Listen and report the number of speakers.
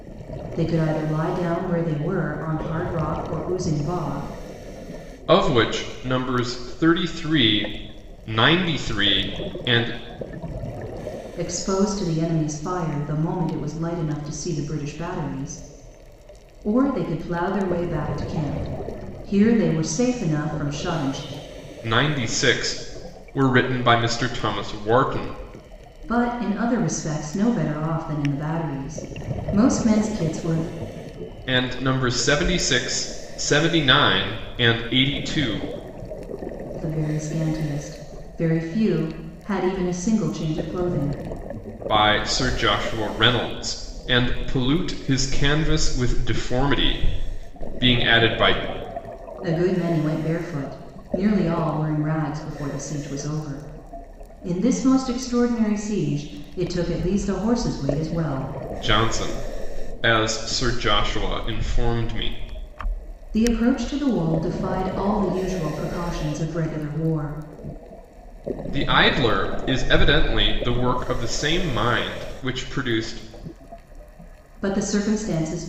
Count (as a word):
two